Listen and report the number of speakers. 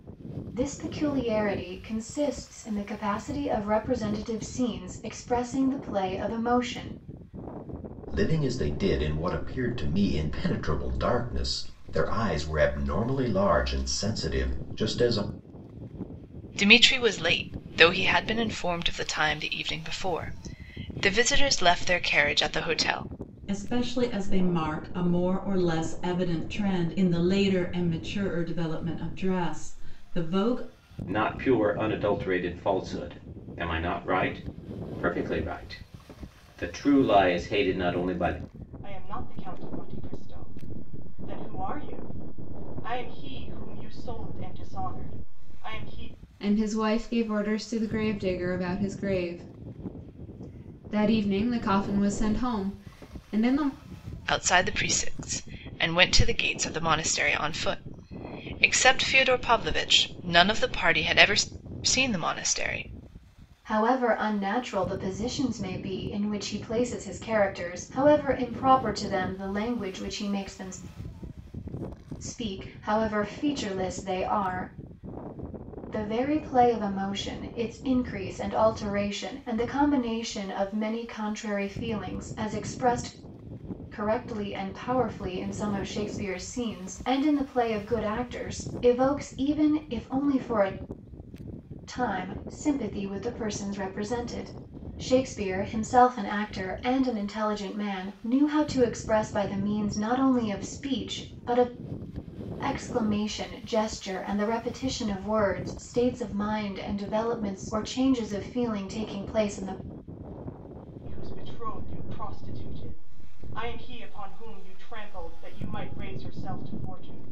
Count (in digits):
7